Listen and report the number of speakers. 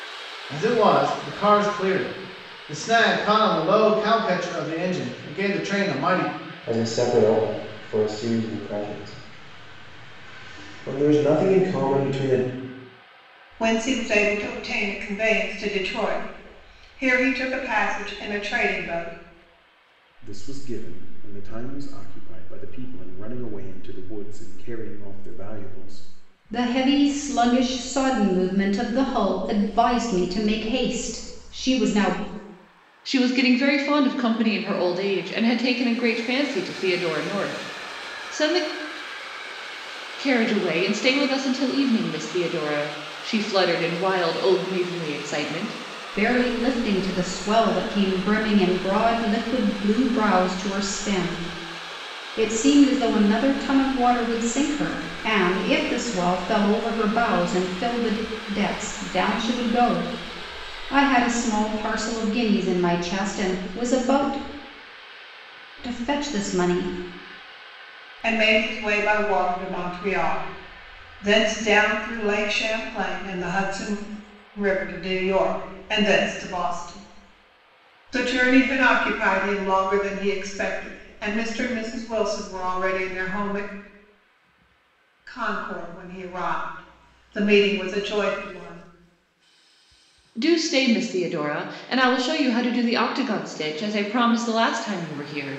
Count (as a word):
six